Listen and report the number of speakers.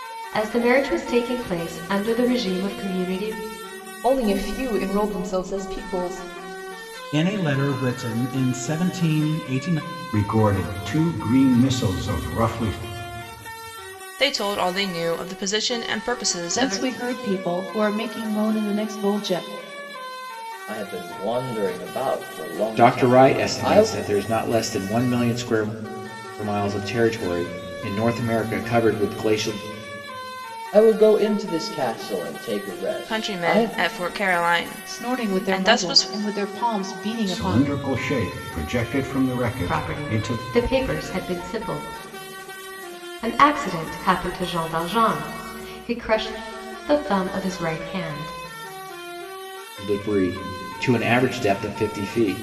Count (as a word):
eight